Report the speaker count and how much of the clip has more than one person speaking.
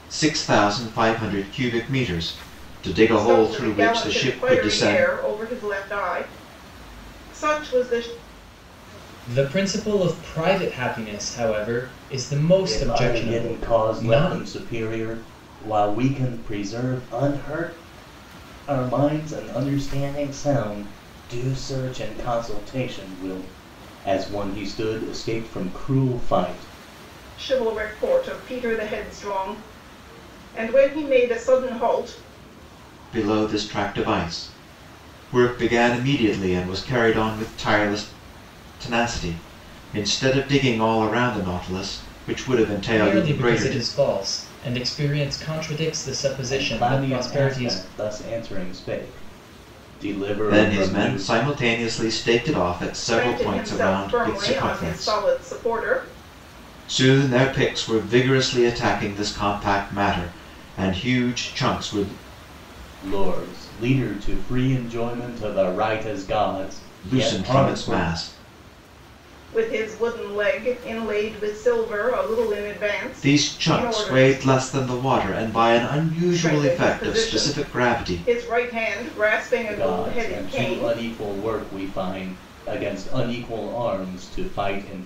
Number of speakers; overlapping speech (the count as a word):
four, about 17%